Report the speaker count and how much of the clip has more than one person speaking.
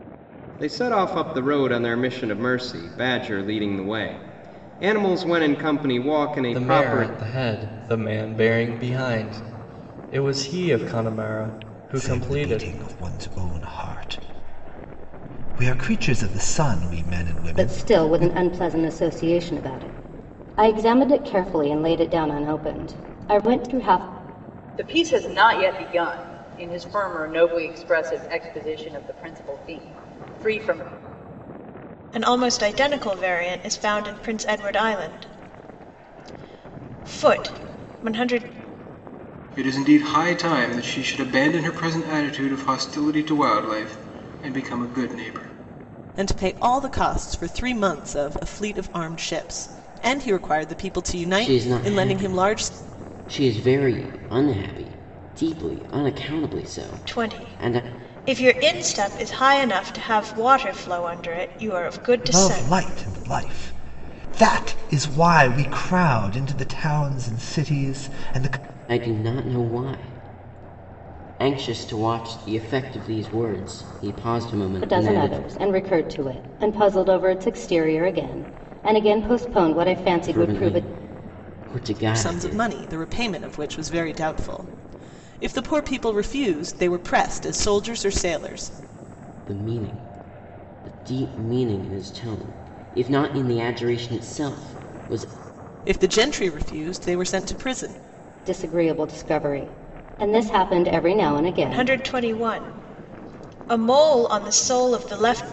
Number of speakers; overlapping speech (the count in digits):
9, about 7%